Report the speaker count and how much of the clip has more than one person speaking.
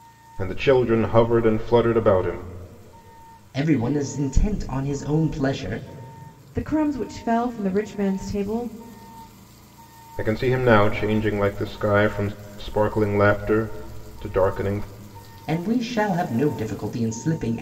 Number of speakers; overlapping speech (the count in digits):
3, no overlap